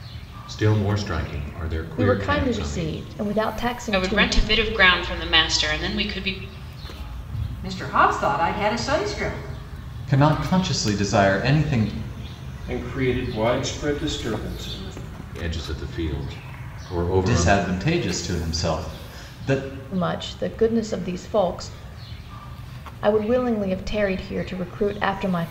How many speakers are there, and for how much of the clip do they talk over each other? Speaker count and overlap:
6, about 7%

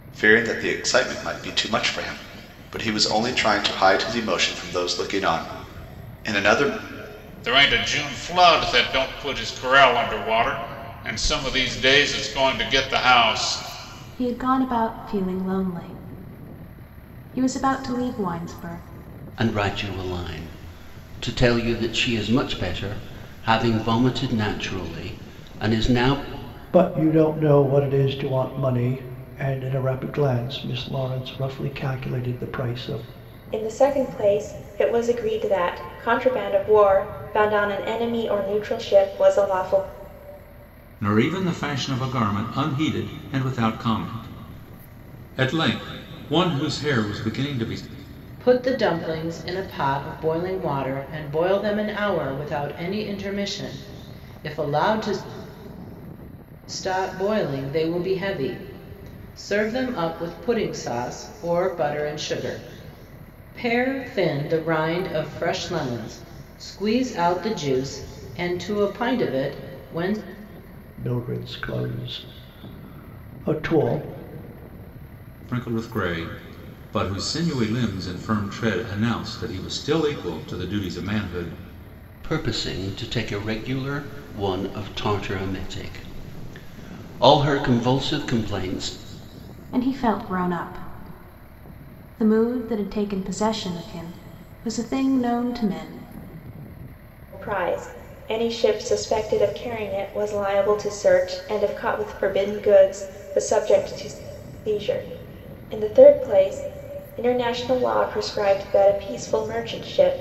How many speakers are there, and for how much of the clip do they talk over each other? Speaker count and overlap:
8, no overlap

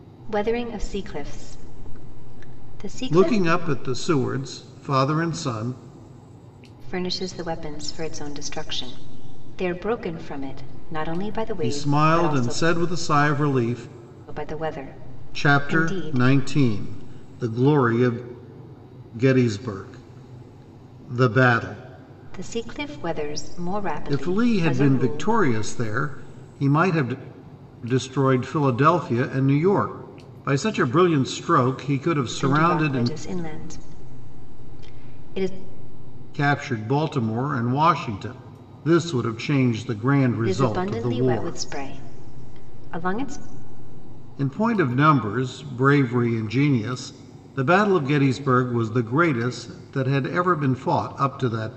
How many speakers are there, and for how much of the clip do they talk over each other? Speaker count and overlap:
2, about 11%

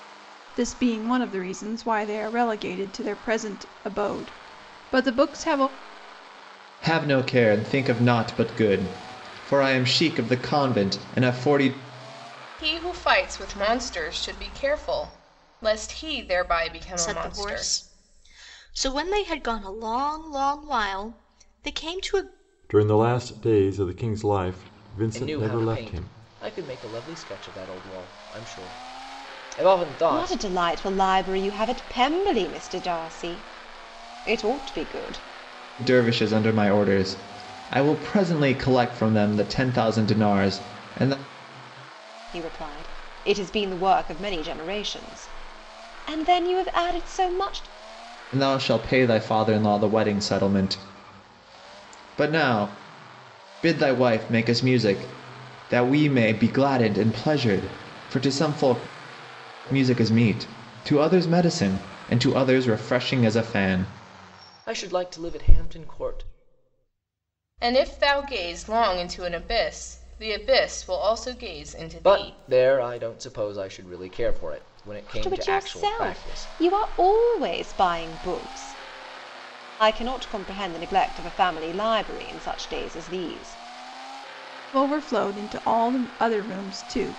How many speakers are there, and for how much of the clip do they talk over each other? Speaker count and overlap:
7, about 5%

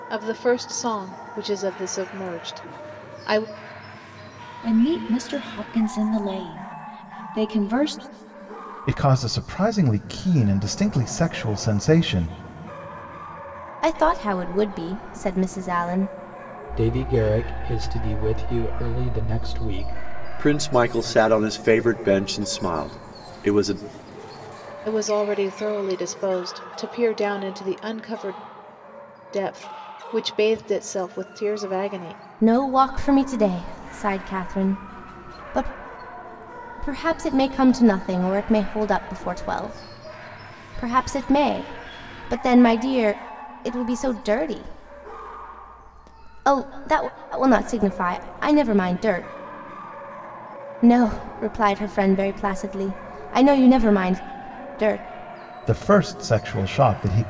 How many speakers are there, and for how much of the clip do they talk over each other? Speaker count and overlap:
6, no overlap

